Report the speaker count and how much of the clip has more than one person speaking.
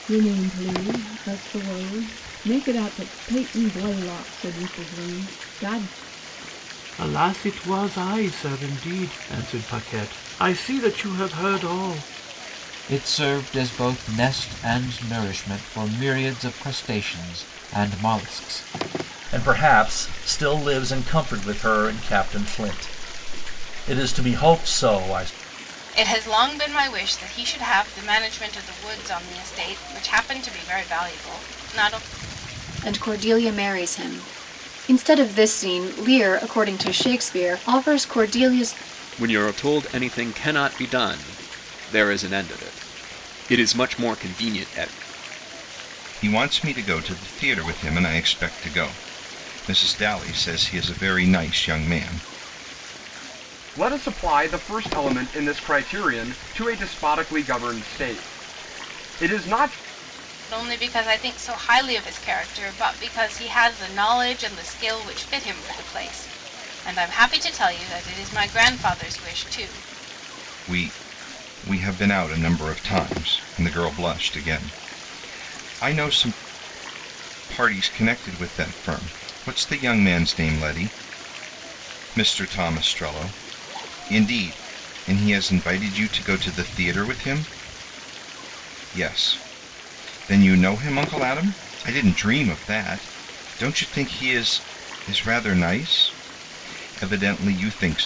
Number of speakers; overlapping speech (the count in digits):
9, no overlap